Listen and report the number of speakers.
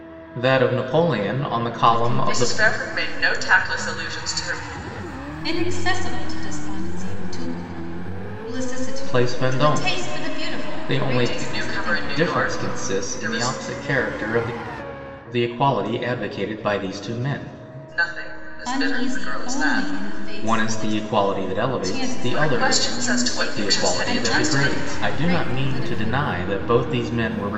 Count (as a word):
three